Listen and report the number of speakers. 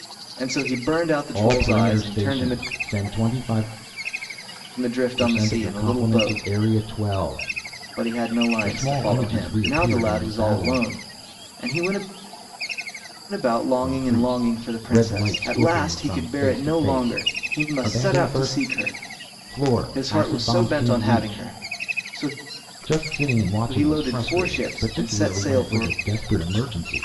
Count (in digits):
2